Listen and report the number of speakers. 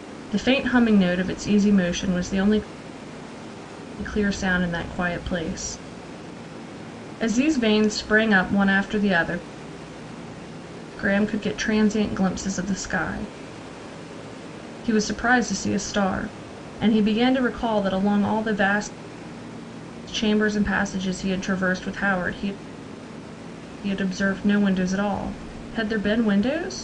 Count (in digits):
1